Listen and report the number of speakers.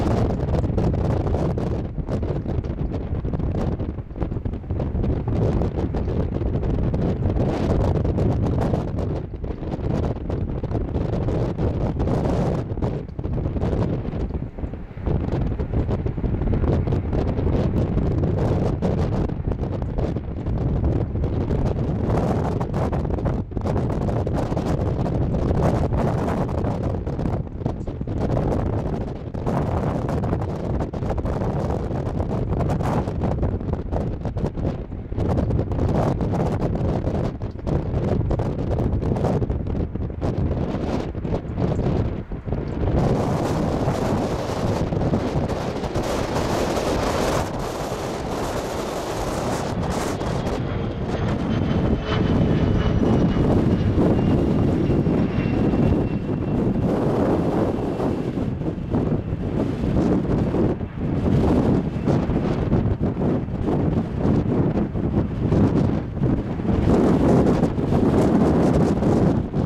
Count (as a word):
zero